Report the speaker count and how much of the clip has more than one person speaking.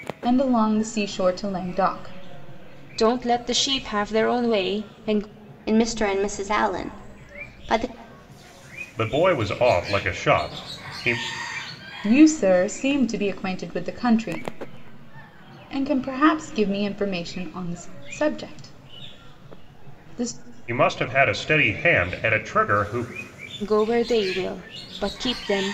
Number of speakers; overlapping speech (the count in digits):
4, no overlap